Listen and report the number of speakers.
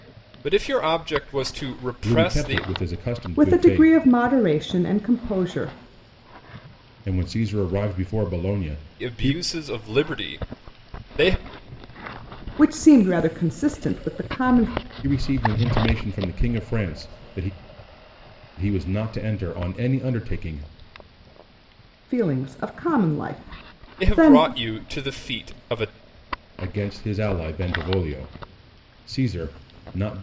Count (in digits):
3